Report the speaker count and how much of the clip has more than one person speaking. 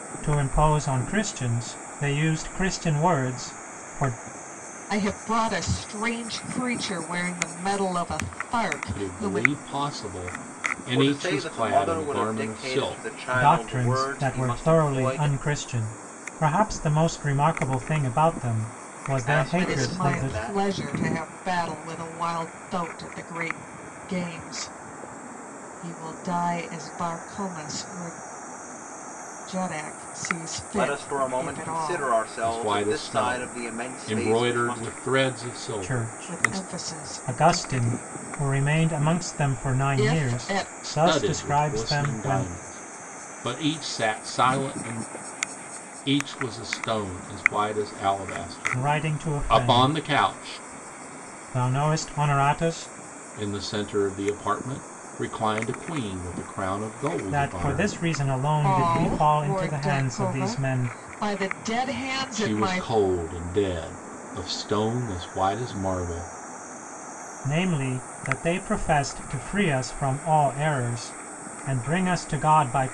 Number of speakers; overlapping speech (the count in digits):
4, about 30%